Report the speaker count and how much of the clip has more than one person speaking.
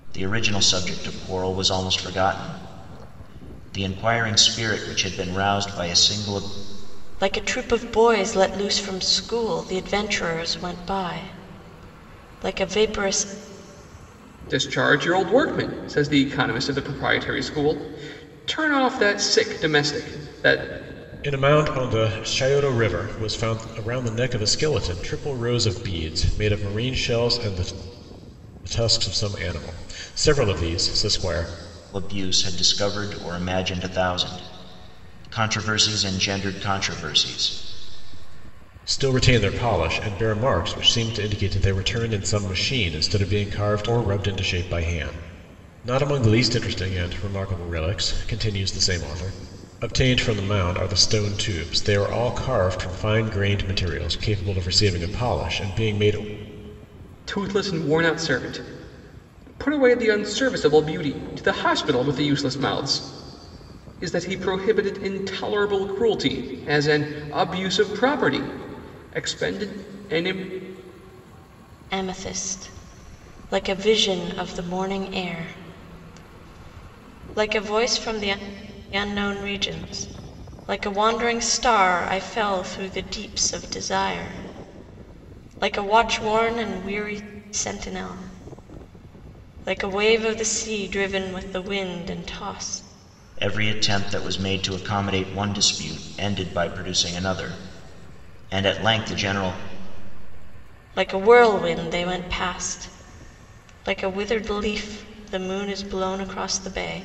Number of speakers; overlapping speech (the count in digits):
4, no overlap